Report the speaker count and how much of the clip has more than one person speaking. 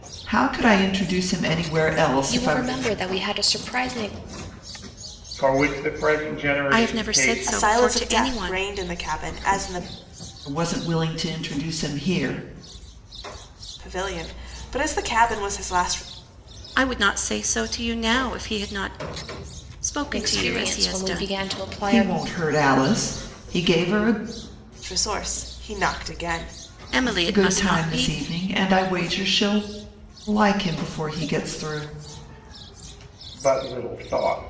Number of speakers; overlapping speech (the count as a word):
five, about 14%